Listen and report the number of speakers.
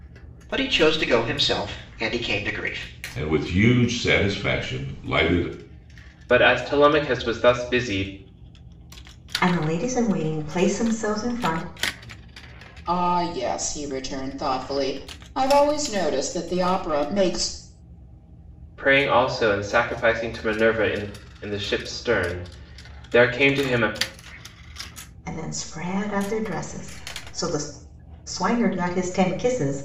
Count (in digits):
5